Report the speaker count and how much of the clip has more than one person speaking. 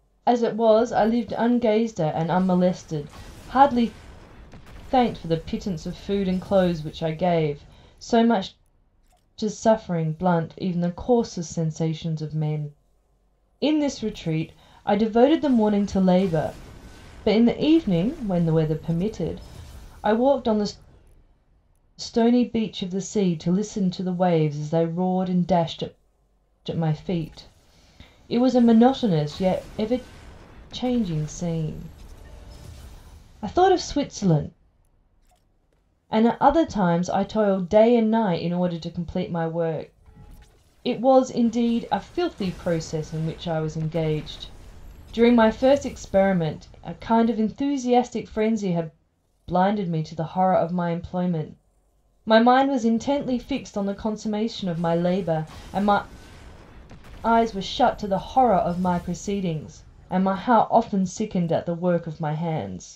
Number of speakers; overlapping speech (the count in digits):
1, no overlap